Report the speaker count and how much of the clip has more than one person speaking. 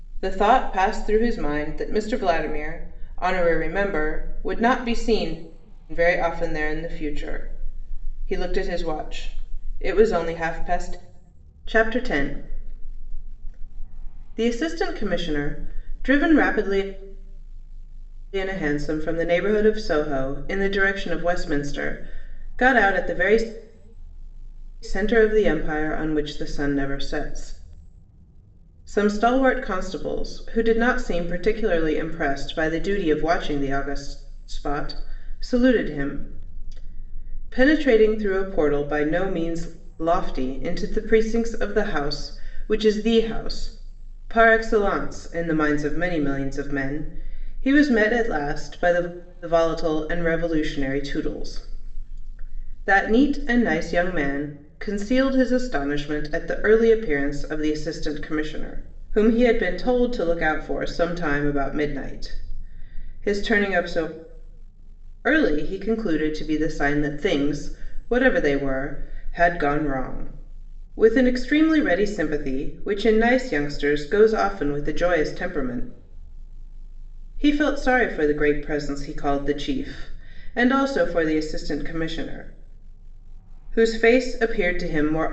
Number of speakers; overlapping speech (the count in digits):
1, no overlap